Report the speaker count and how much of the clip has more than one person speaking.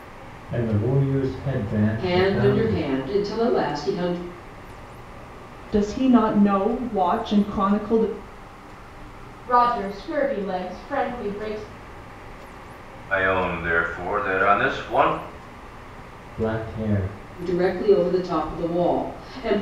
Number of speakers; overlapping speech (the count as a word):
five, about 5%